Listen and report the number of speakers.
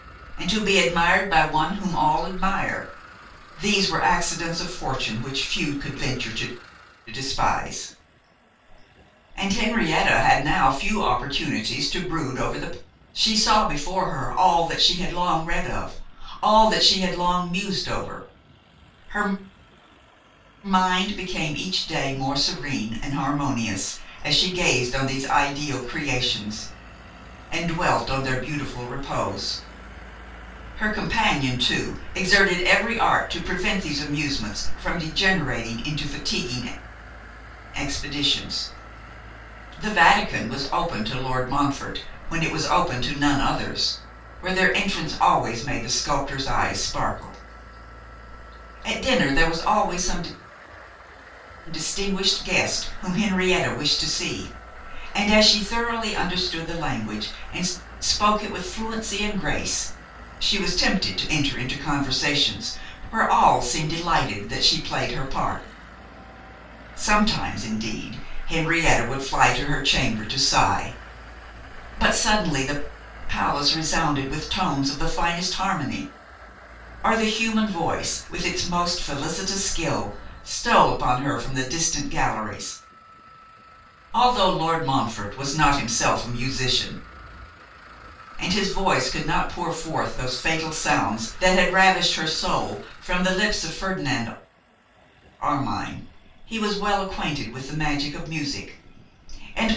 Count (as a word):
one